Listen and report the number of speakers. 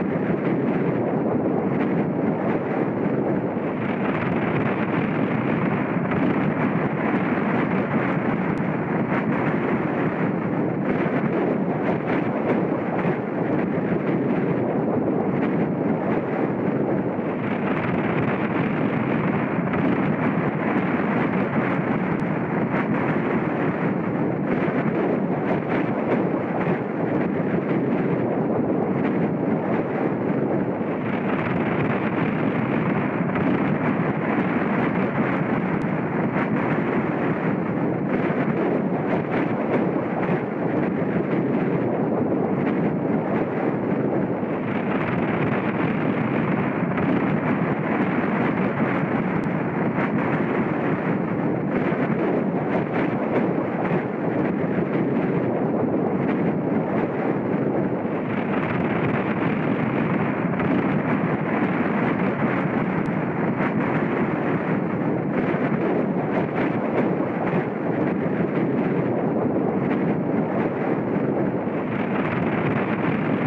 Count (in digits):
0